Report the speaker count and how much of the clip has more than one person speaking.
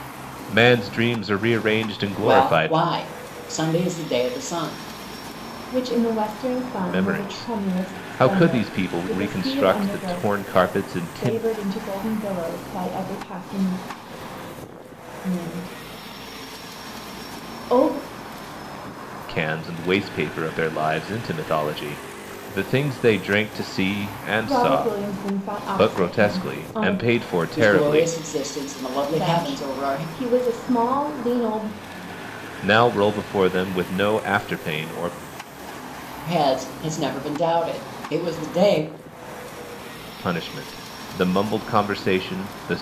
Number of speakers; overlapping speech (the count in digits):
3, about 18%